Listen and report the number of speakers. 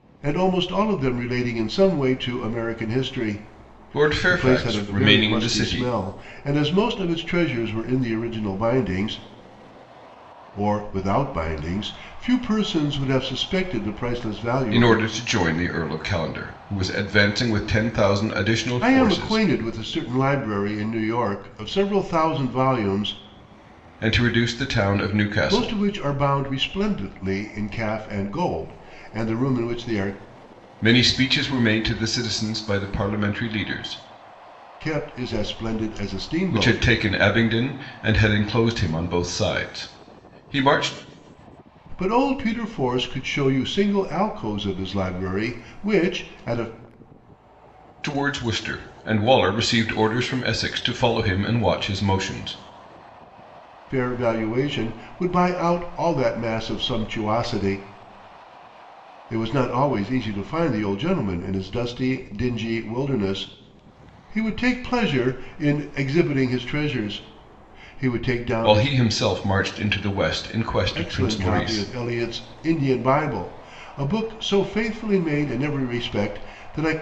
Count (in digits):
2